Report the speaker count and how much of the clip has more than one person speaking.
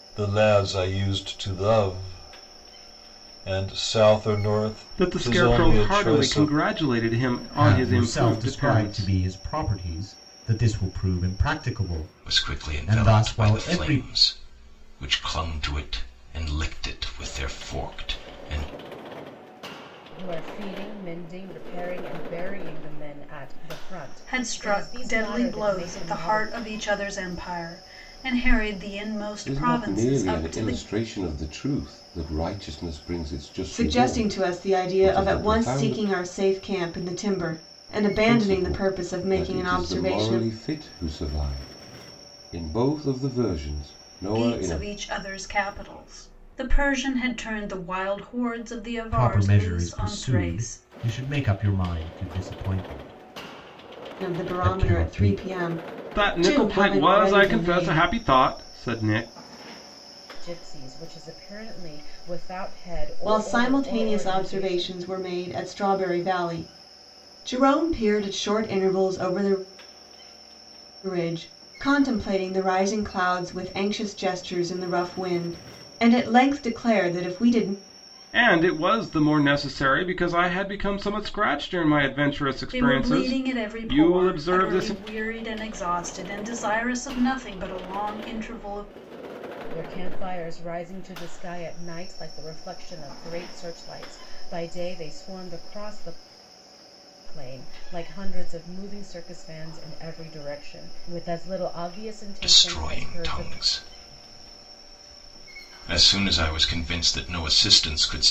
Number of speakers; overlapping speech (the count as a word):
eight, about 22%